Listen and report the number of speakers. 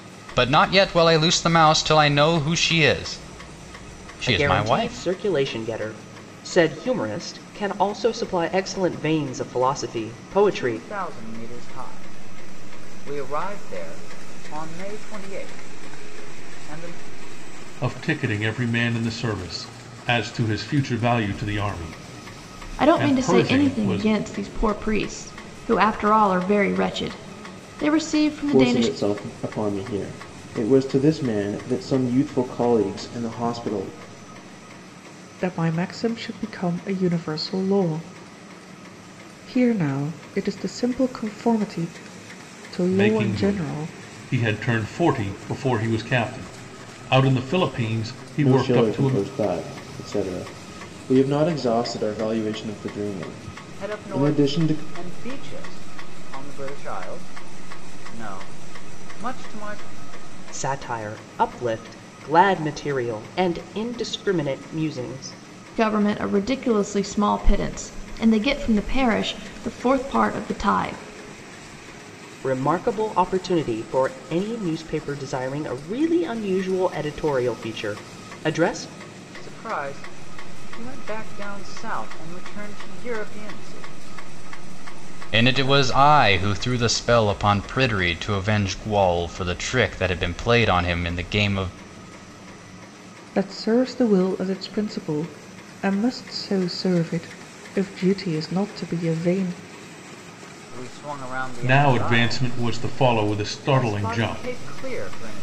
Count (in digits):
7